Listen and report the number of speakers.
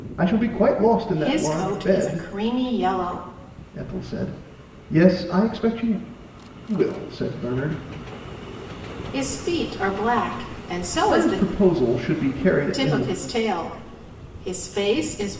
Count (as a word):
two